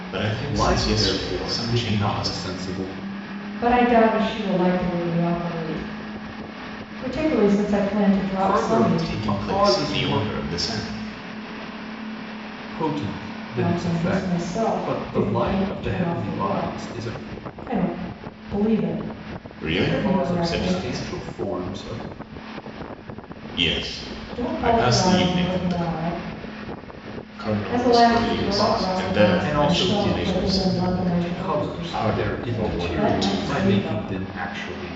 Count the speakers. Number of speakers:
three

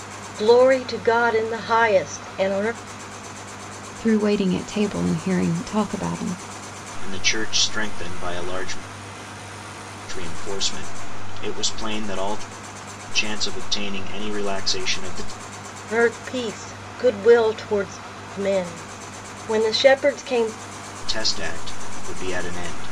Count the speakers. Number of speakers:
three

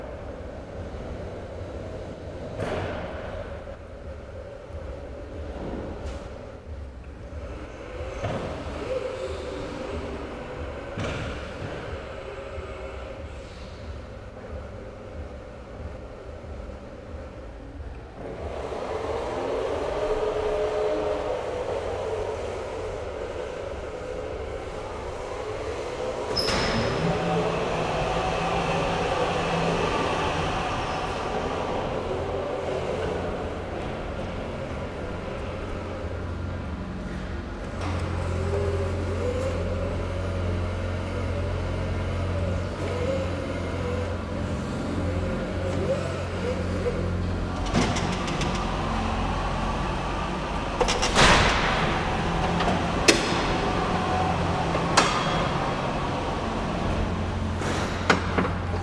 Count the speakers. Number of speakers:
zero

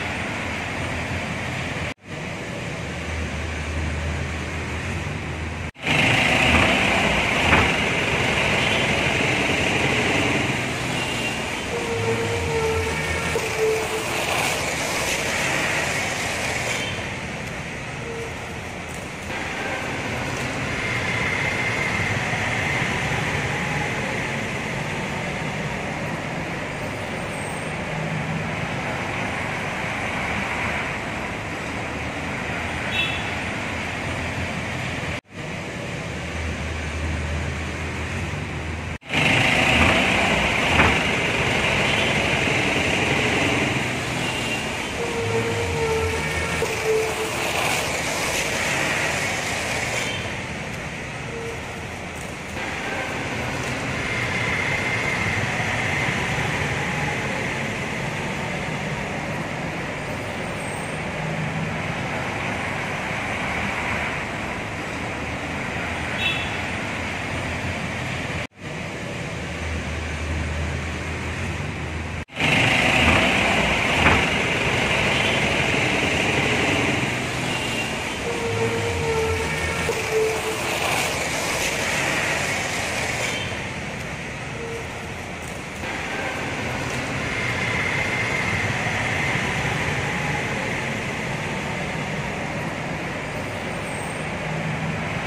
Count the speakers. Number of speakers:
zero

